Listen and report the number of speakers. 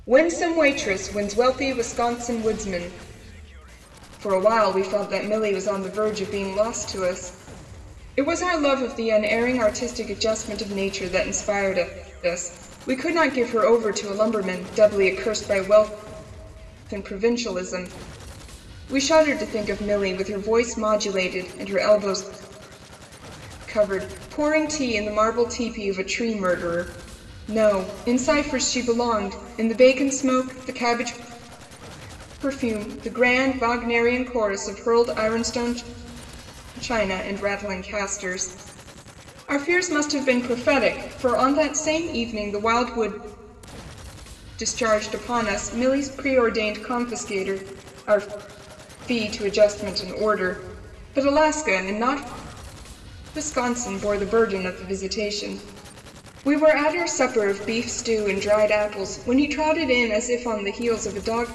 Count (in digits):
1